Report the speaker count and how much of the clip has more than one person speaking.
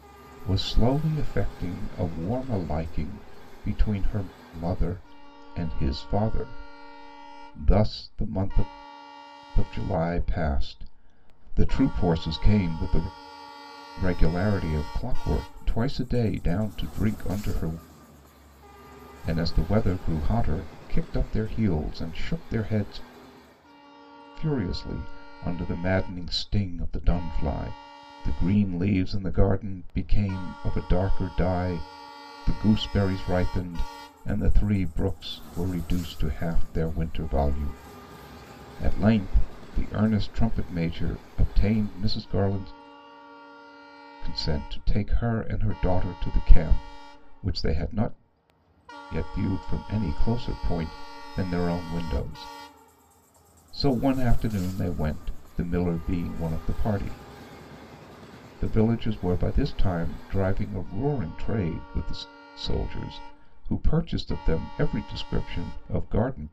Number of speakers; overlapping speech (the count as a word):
one, no overlap